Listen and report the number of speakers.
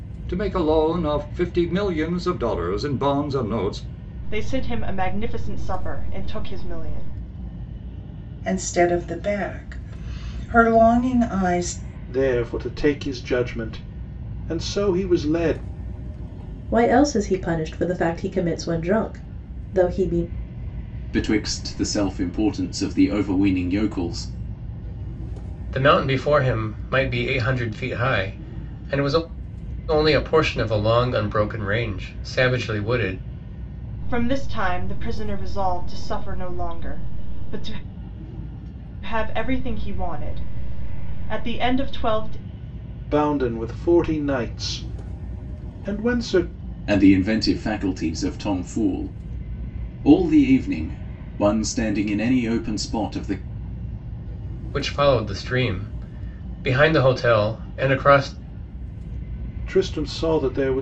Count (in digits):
7